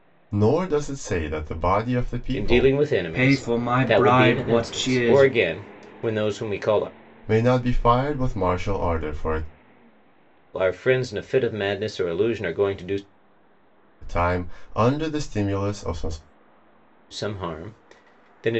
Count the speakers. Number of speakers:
three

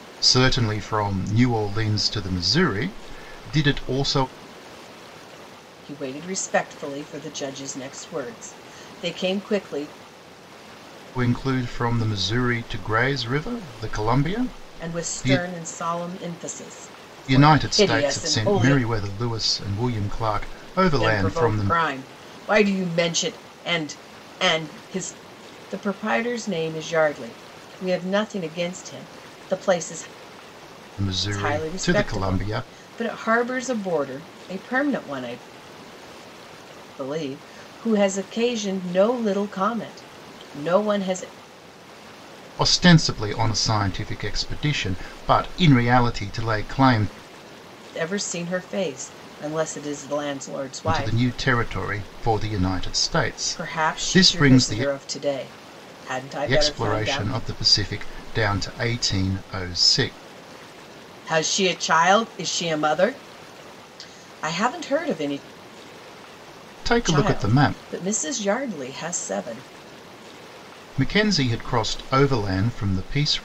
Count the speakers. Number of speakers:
two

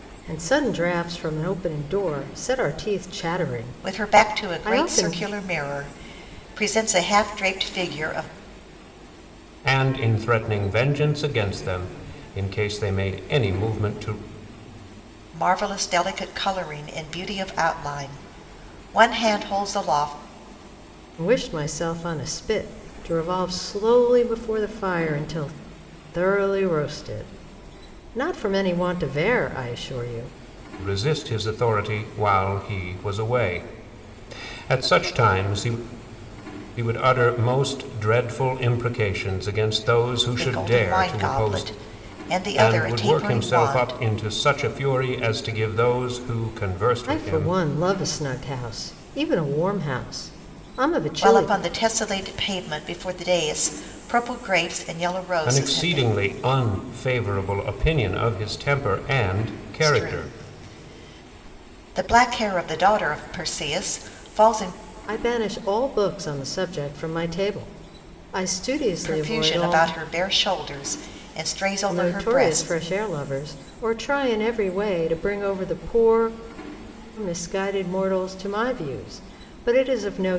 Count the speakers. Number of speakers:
three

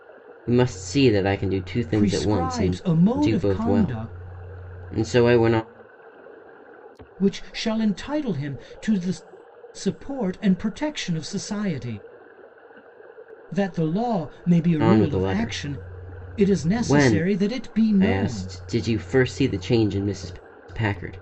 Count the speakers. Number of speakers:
two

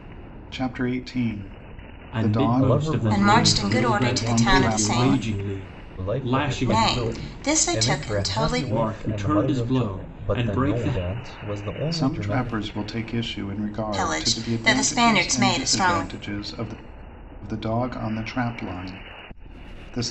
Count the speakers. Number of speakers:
four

